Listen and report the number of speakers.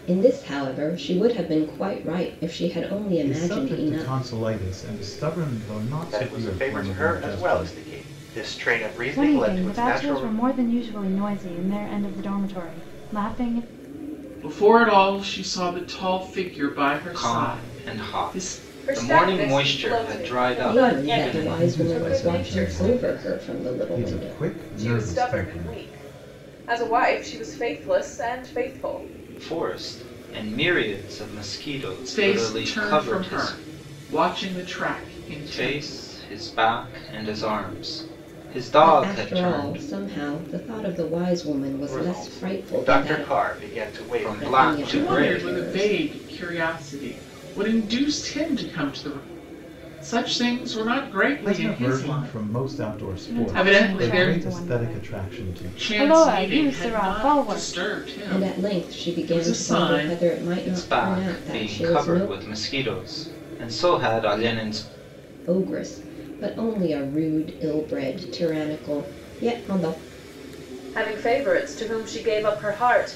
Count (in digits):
7